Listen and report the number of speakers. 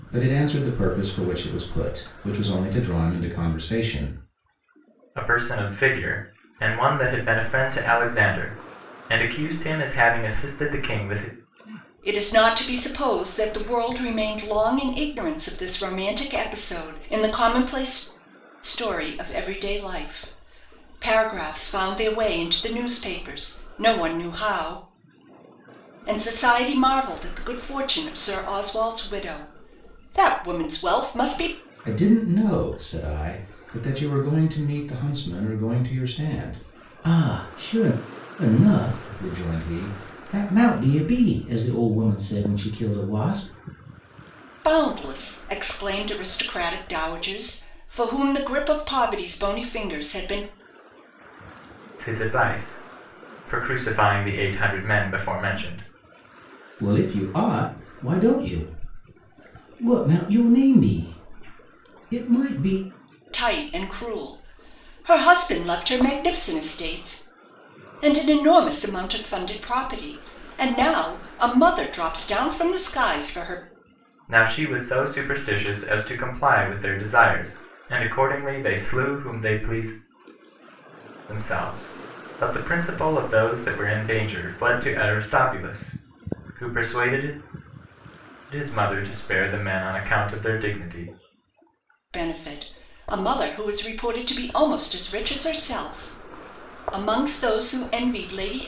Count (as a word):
three